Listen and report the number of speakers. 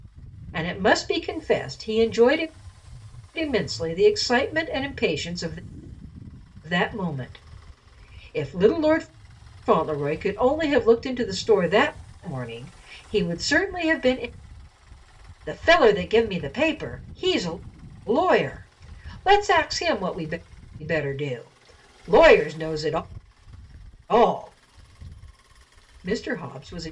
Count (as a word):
one